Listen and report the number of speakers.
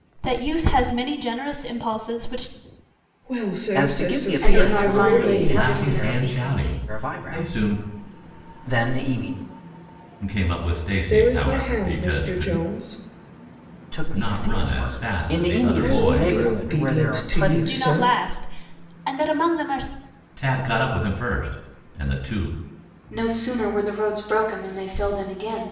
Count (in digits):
5